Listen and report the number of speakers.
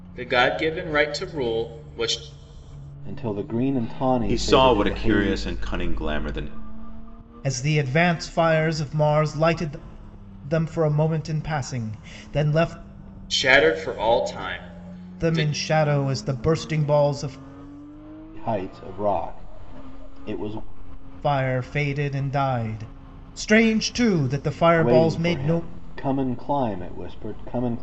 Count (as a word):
four